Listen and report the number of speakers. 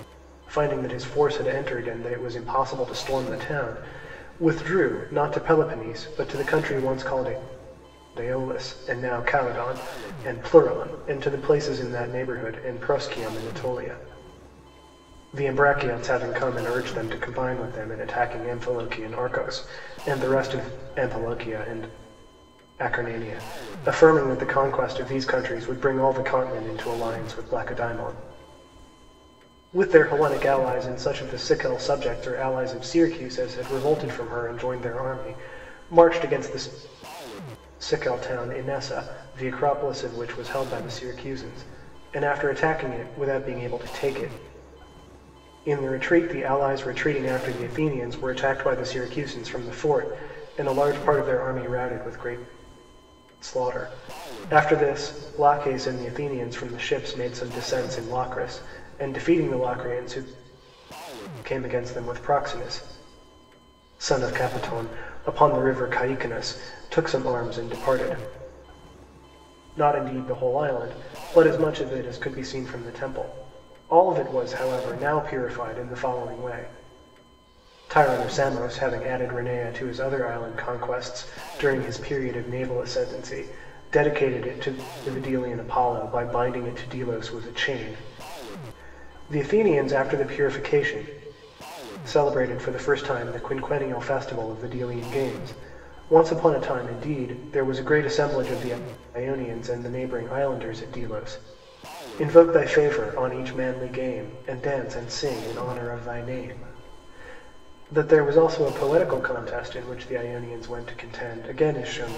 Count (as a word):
one